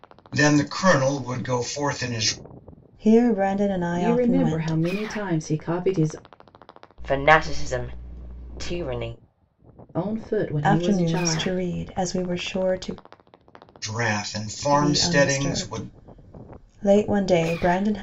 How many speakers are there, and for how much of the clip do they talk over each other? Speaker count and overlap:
four, about 17%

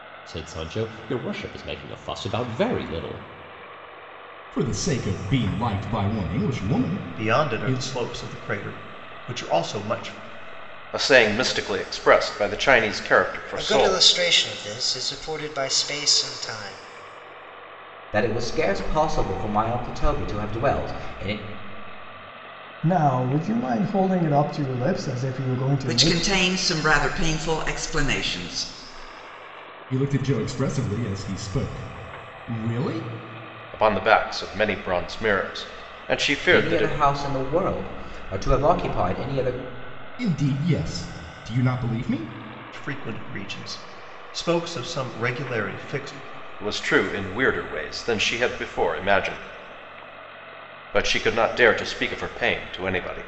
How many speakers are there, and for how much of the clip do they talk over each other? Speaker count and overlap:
eight, about 4%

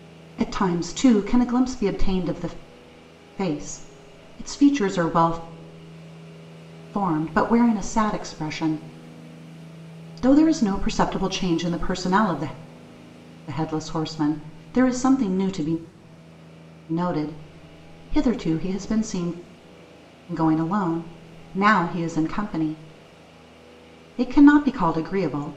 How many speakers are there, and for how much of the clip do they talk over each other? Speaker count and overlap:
one, no overlap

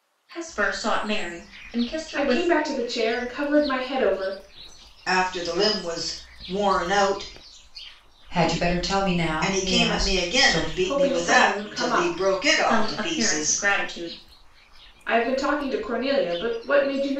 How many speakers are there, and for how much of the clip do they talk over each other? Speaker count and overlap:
four, about 24%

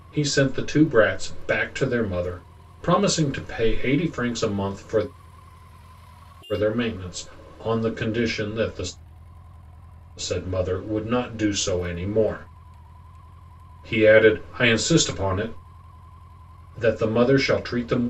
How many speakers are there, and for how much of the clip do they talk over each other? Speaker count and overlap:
one, no overlap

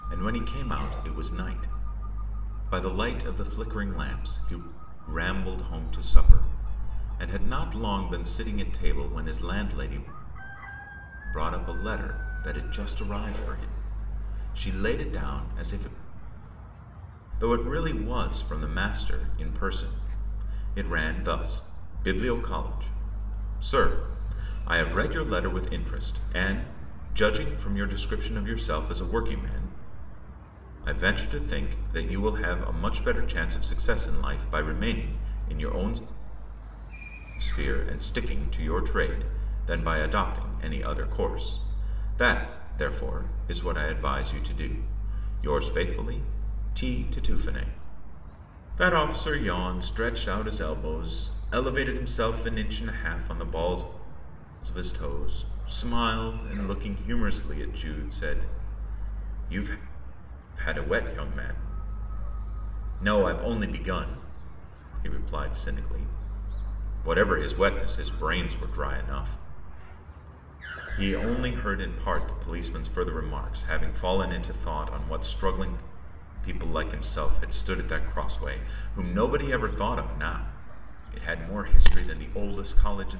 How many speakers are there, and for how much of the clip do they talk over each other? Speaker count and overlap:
one, no overlap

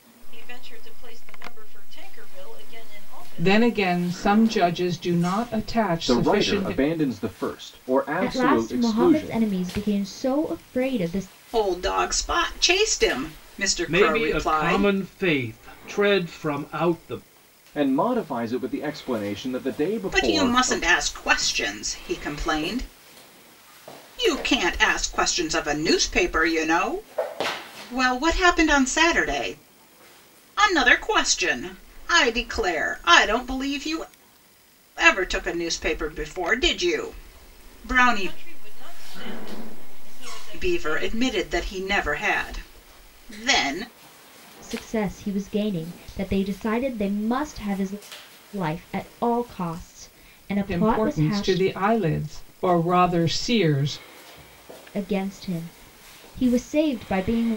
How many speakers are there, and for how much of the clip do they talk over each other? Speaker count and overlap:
six, about 11%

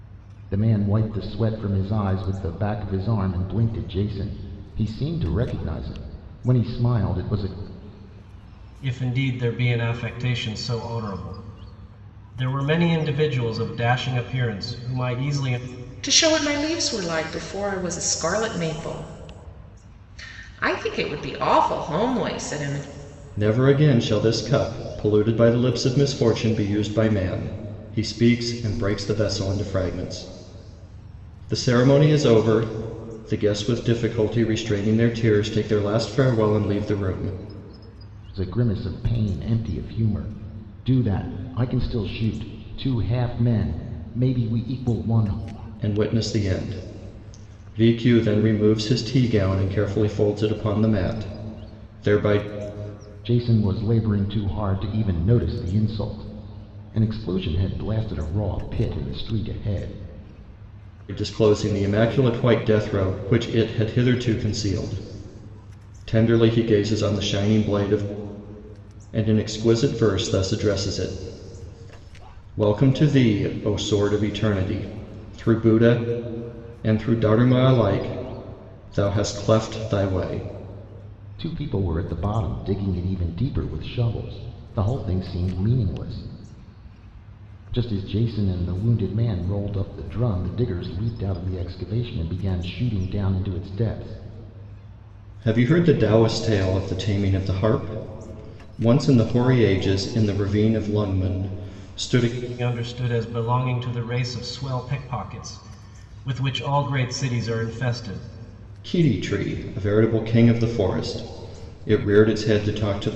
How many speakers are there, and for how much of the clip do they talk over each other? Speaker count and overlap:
four, no overlap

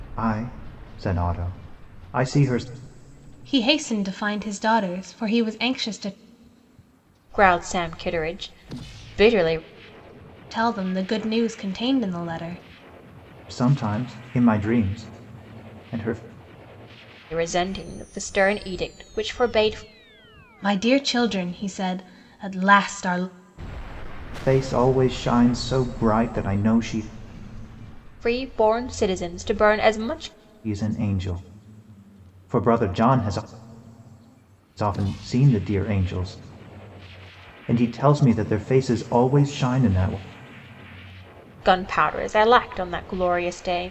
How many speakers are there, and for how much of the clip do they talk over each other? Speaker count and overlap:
three, no overlap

